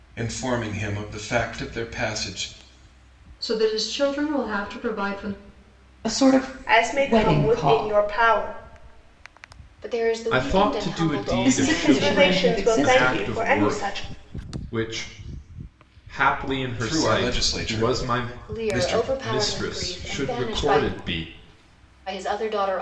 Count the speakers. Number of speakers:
six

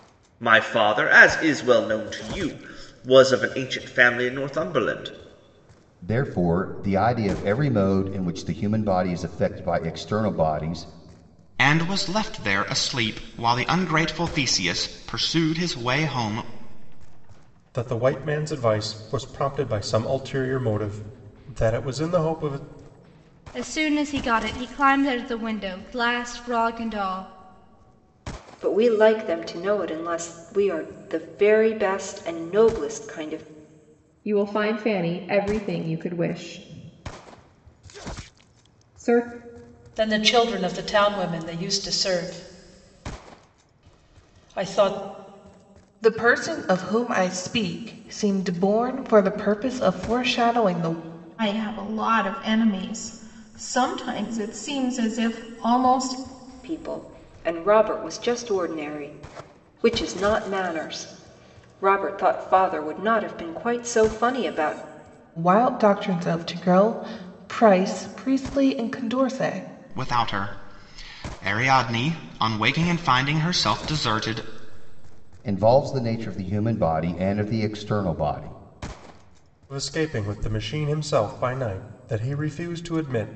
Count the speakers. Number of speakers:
ten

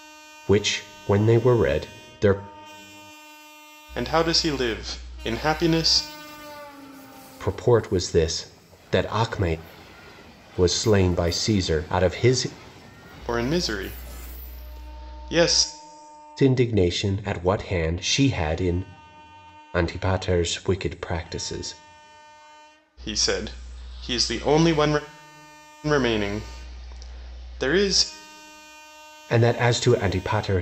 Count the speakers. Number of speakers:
two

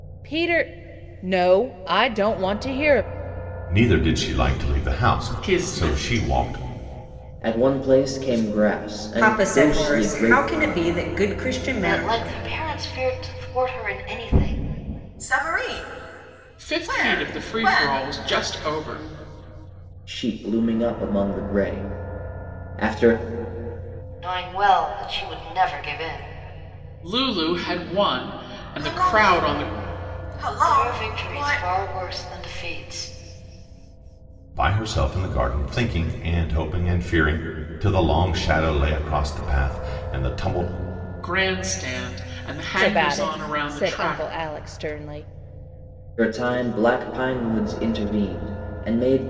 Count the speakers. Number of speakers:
seven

